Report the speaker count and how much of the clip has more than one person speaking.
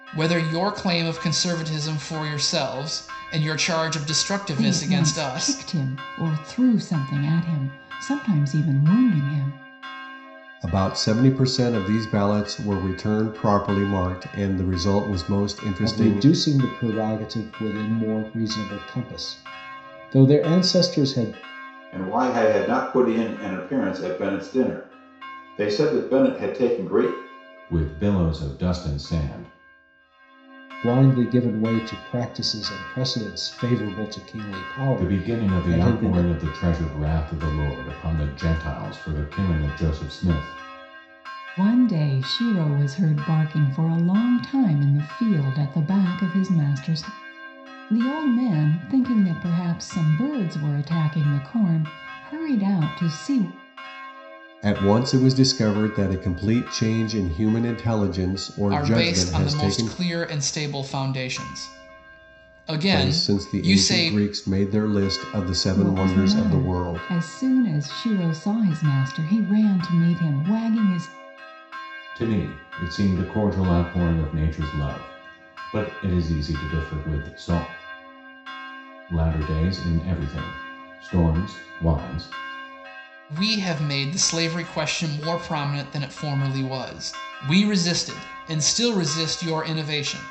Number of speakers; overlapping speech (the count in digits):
6, about 8%